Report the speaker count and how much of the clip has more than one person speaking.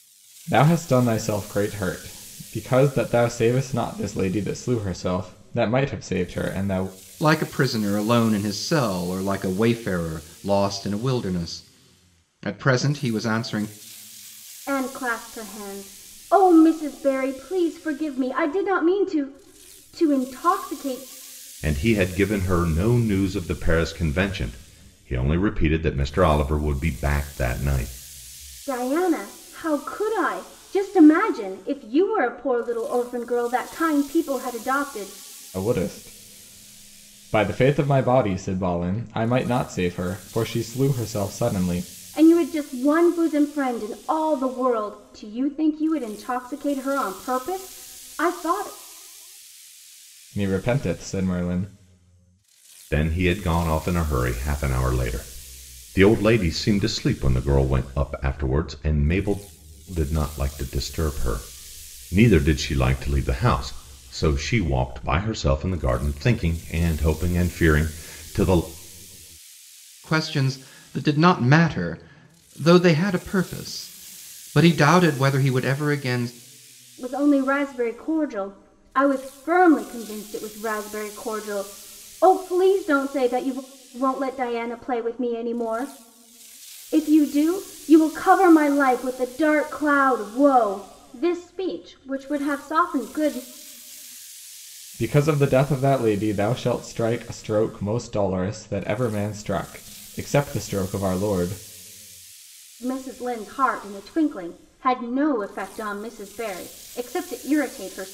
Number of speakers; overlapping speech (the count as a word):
four, no overlap